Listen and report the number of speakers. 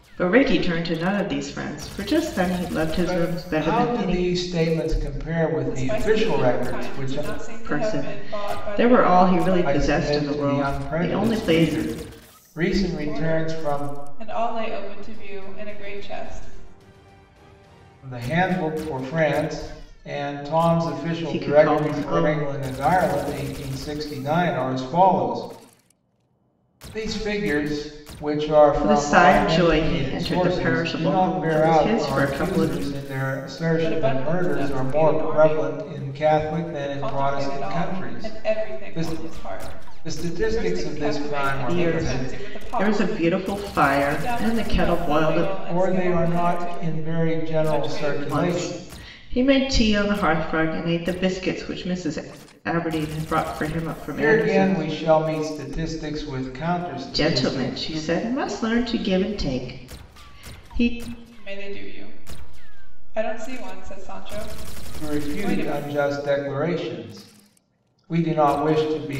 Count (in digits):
3